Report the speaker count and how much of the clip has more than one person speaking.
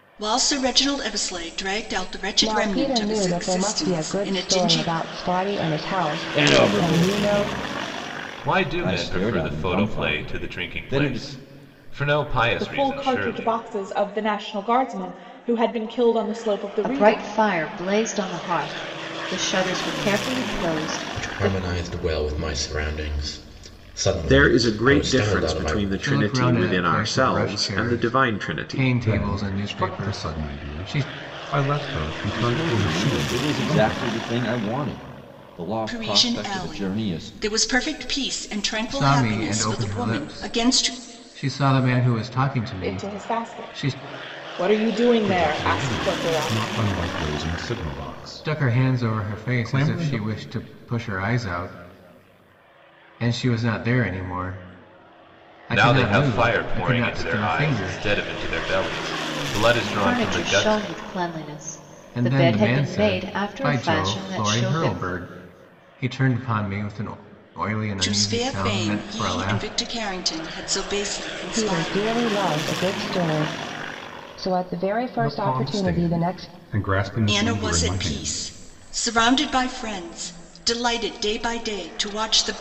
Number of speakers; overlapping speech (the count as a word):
ten, about 44%